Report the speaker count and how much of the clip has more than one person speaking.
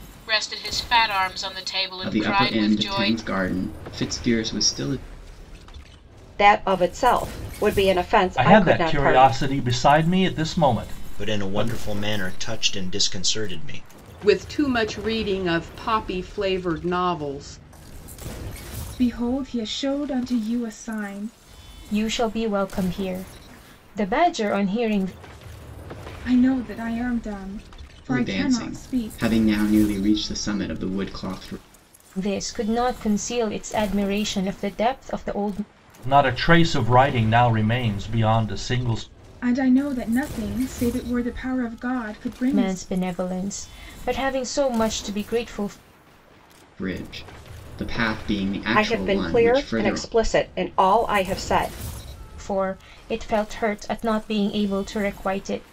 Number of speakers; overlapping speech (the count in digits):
8, about 10%